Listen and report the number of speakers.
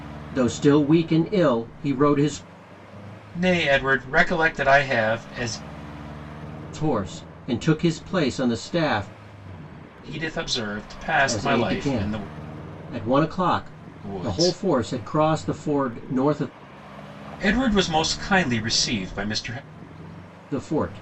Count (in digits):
2